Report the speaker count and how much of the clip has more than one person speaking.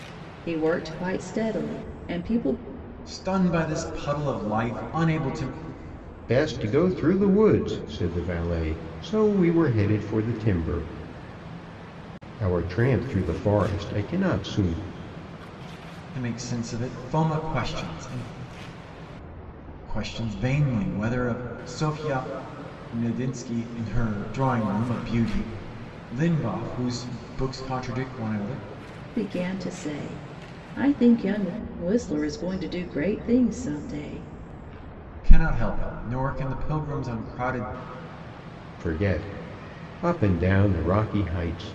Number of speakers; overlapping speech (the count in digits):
3, no overlap